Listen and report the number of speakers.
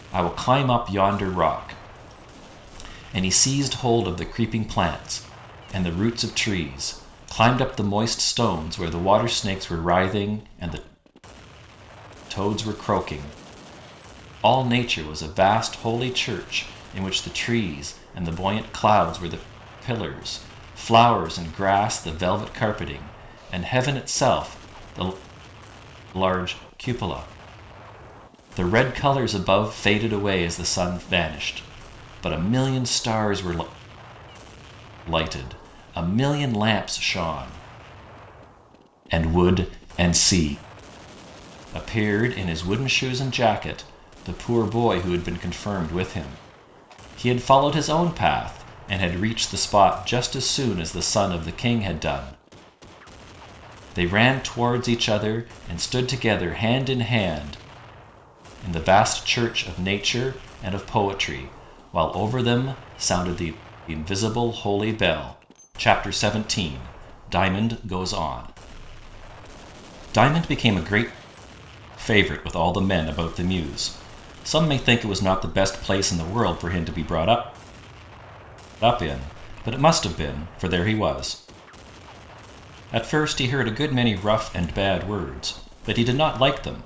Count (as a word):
one